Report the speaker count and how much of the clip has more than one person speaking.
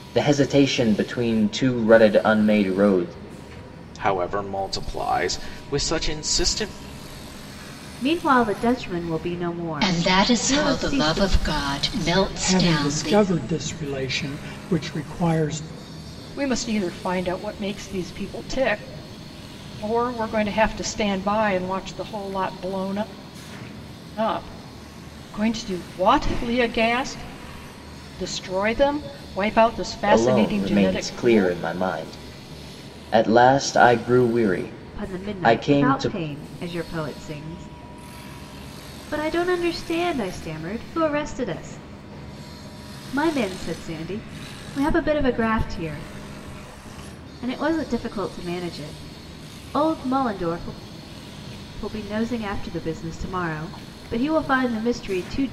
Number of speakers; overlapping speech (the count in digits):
6, about 9%